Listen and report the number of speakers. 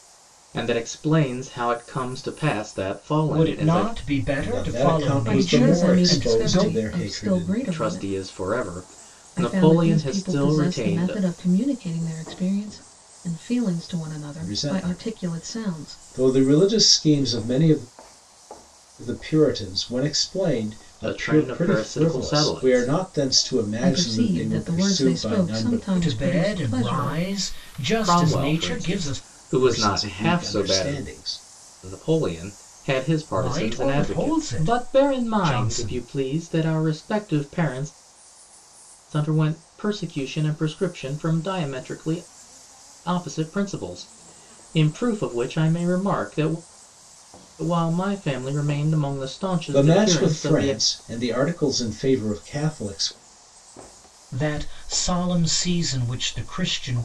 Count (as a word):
four